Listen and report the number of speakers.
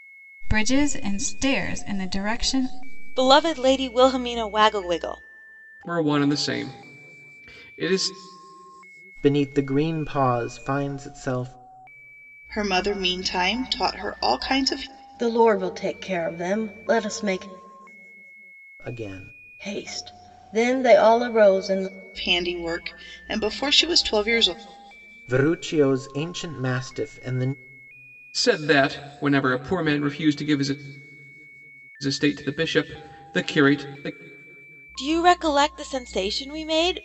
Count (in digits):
6